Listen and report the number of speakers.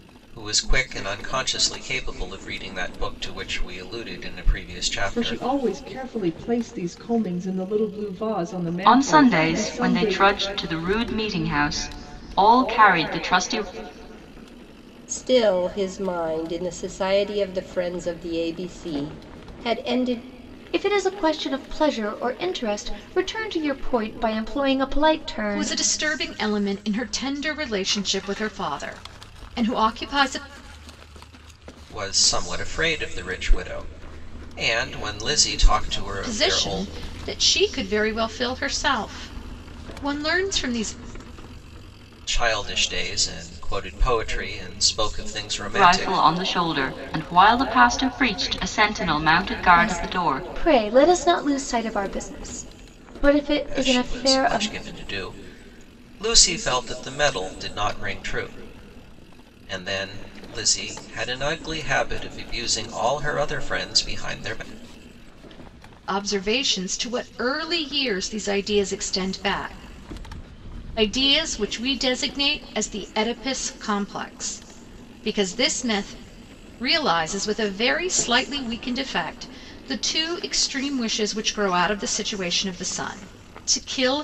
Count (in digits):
6